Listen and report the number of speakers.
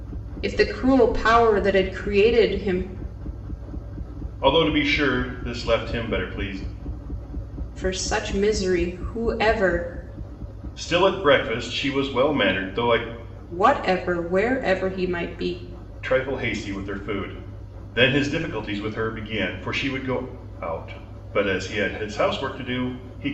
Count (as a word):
two